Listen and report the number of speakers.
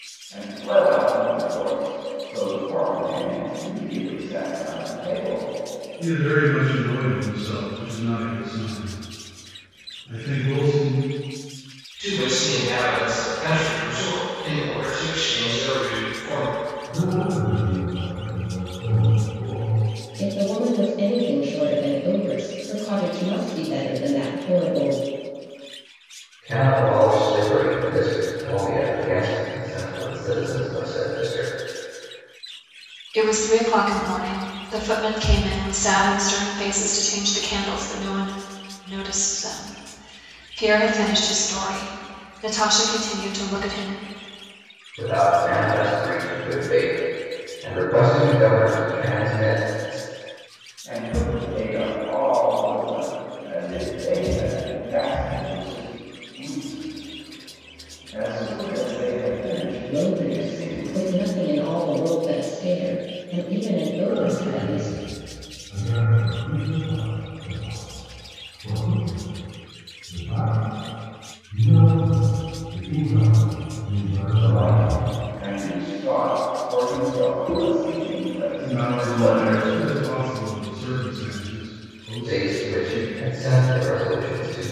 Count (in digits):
7